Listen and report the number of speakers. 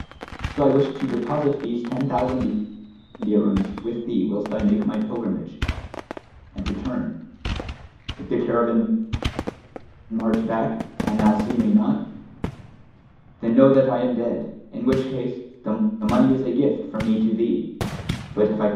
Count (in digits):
1